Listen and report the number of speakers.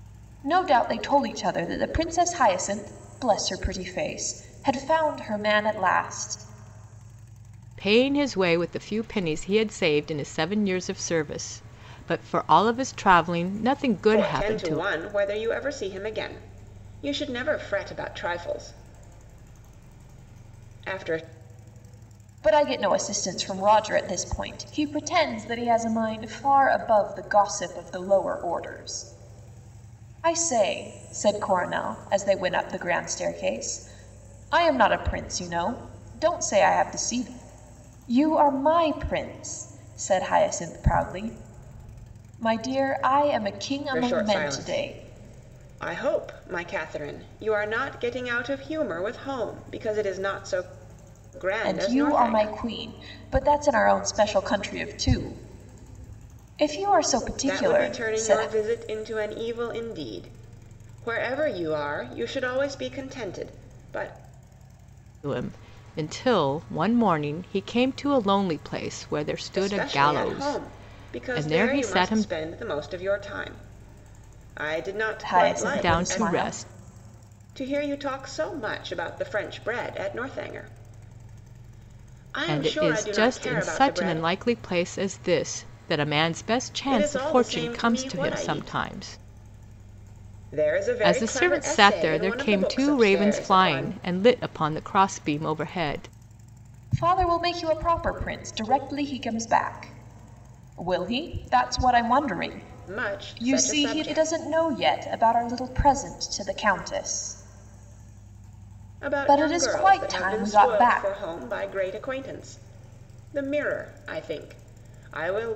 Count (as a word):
three